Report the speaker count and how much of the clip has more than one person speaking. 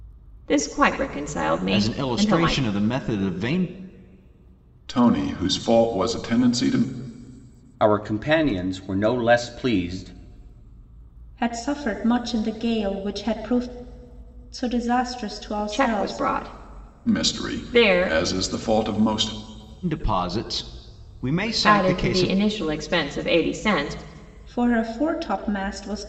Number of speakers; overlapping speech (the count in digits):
5, about 13%